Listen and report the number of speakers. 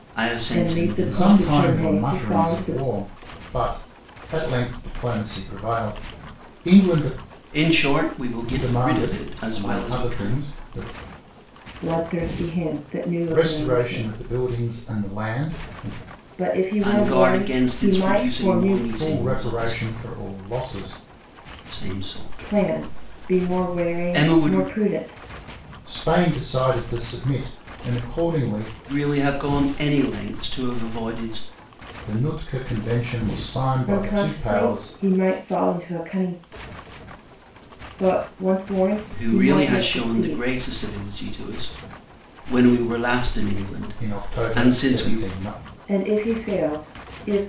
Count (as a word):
three